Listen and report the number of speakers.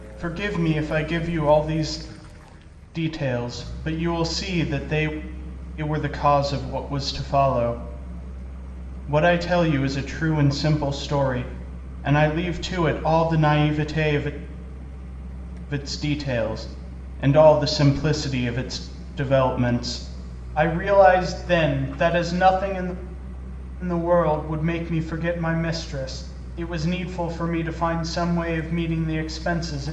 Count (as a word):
one